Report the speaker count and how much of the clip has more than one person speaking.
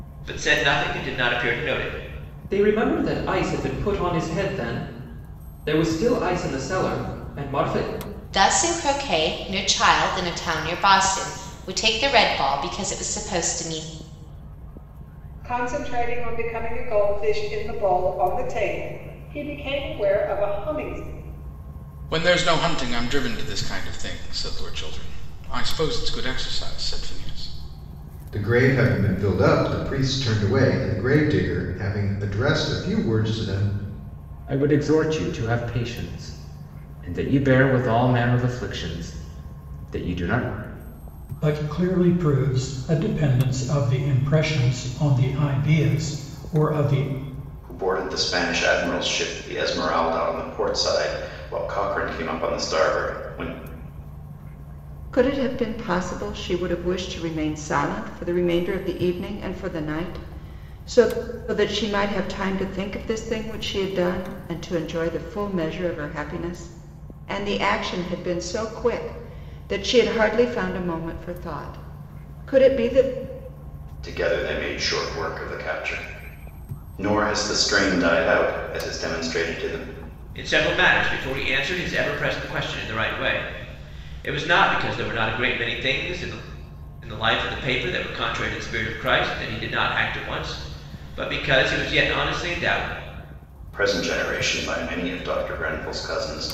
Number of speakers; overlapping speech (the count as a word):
ten, no overlap